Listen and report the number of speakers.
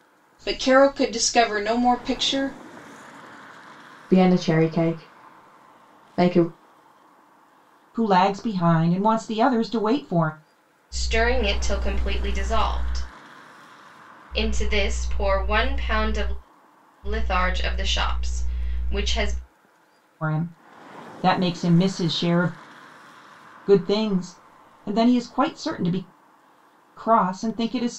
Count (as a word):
four